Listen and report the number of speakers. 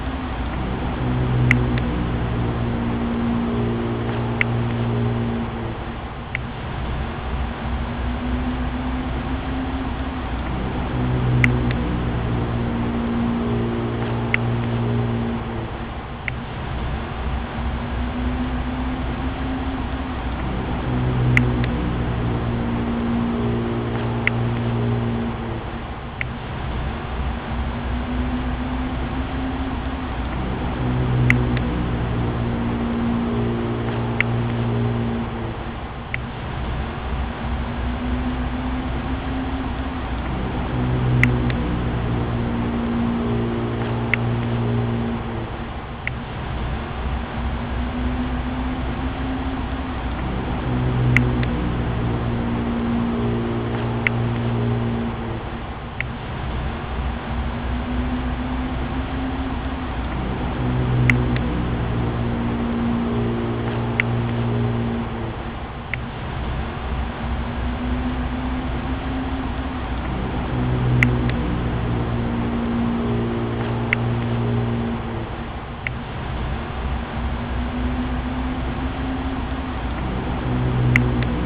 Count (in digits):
0